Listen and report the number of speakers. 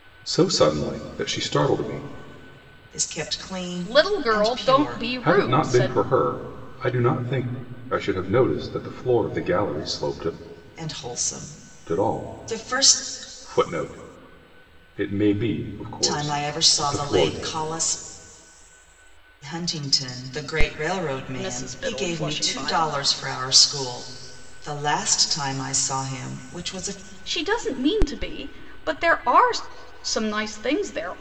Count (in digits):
3